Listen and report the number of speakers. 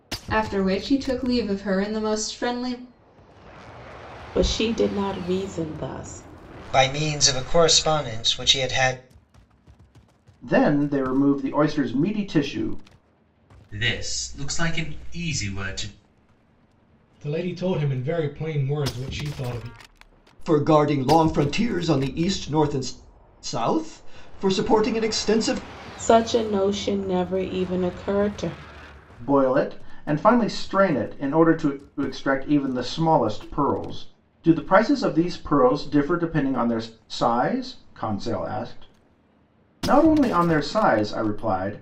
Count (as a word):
seven